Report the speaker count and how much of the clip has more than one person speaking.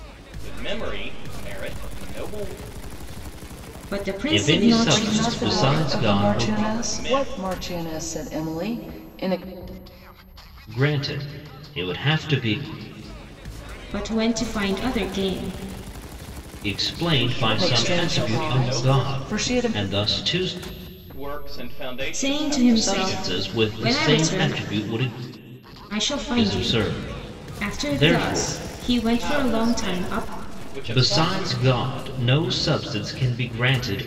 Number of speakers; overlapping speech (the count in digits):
4, about 37%